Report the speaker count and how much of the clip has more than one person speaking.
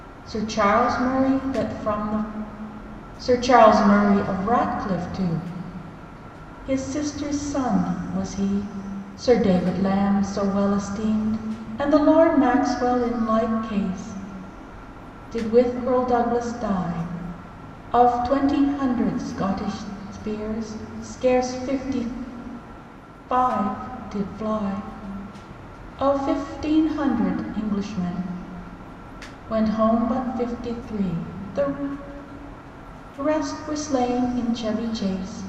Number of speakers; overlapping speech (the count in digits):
1, no overlap